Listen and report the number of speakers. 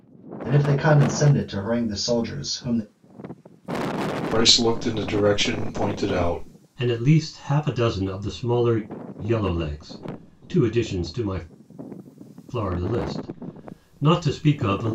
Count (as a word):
three